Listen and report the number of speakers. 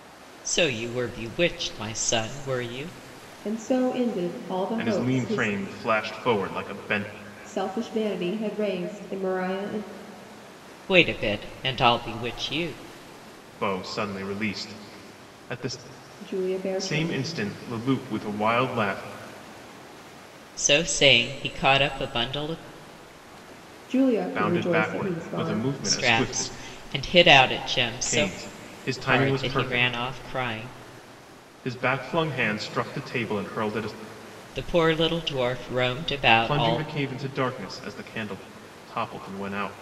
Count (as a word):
three